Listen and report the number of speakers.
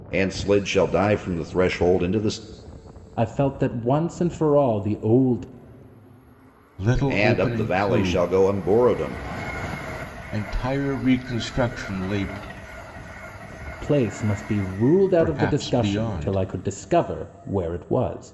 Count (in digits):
3